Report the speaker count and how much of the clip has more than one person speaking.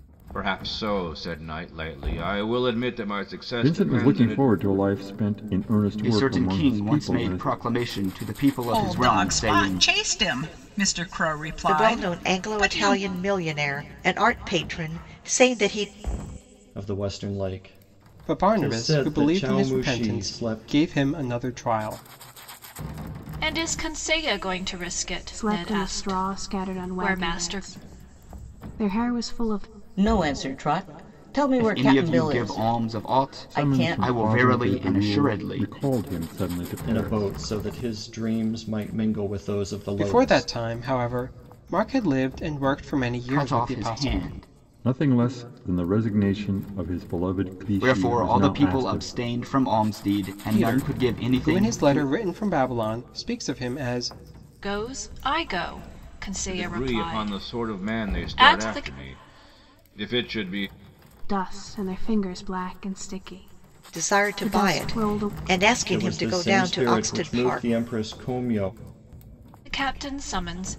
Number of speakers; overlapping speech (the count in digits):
10, about 35%